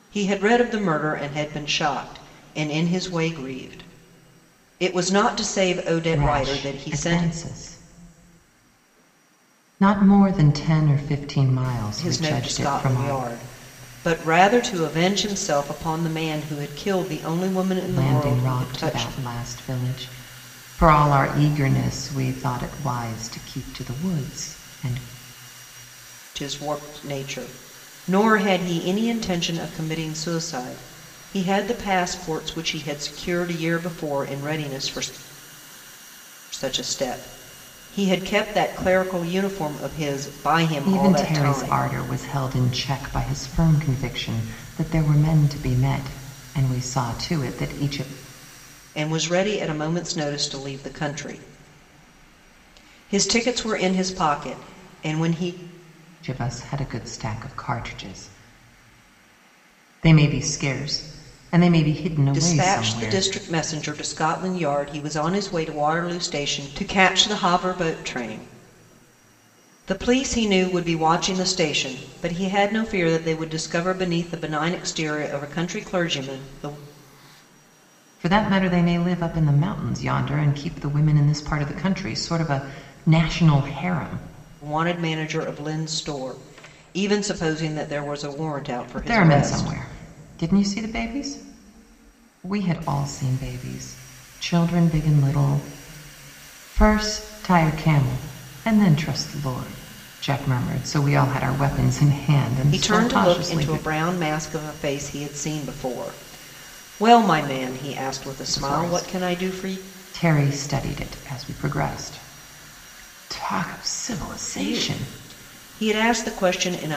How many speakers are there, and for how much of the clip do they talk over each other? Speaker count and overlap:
2, about 8%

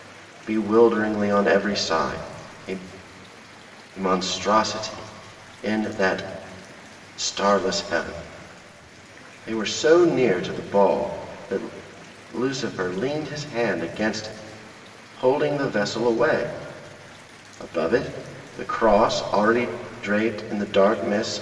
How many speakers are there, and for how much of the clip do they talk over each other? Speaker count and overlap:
1, no overlap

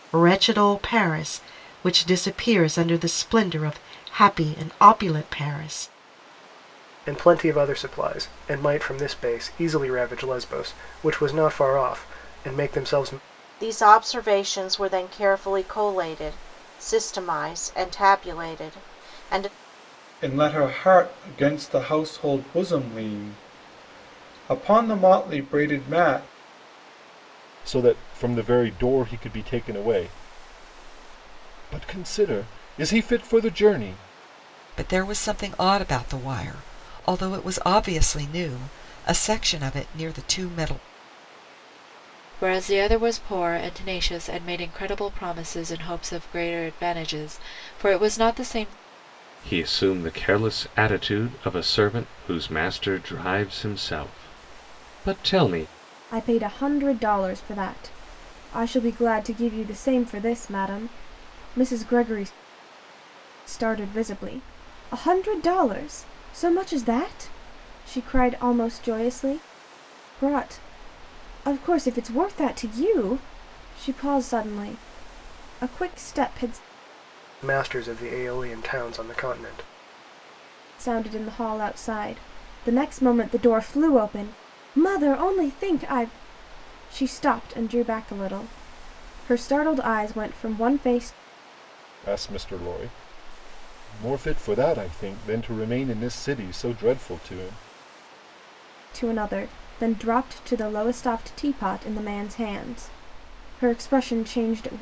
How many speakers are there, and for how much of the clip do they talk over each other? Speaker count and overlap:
9, no overlap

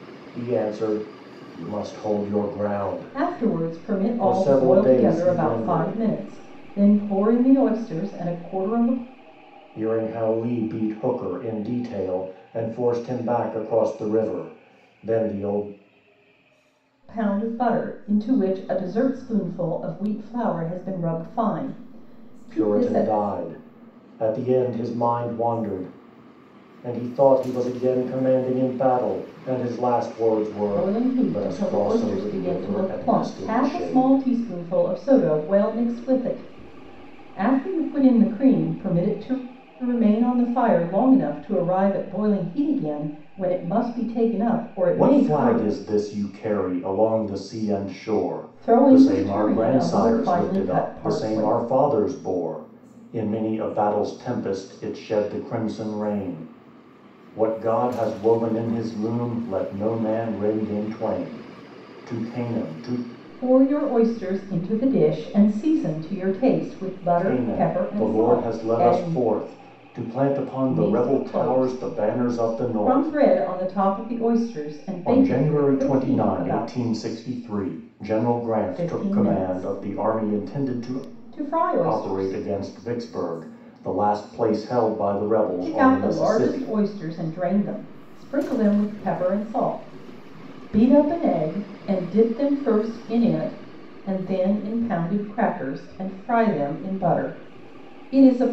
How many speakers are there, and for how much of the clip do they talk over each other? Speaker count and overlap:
2, about 22%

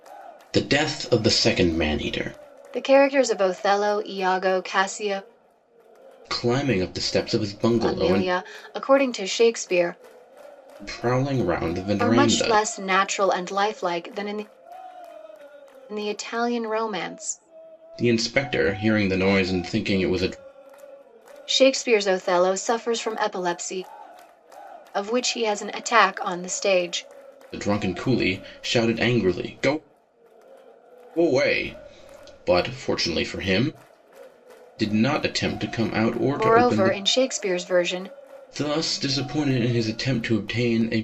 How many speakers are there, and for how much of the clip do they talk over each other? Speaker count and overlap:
2, about 5%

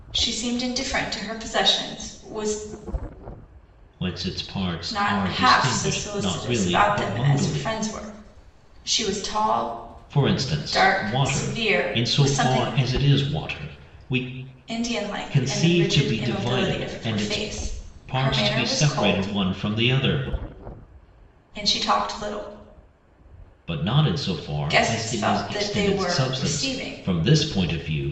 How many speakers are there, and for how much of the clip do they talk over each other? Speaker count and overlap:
2, about 39%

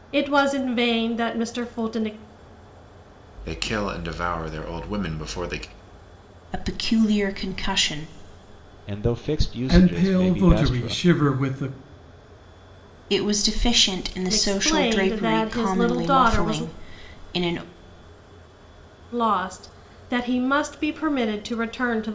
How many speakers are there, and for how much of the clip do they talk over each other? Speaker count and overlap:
5, about 17%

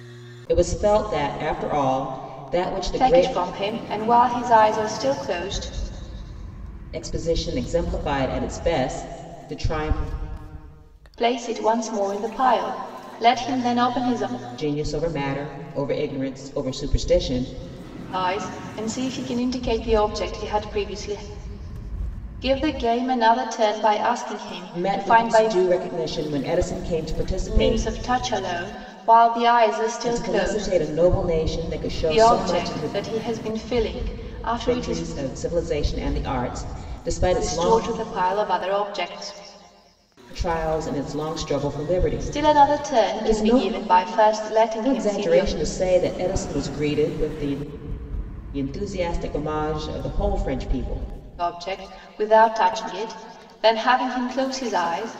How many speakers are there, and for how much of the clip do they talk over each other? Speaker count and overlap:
2, about 12%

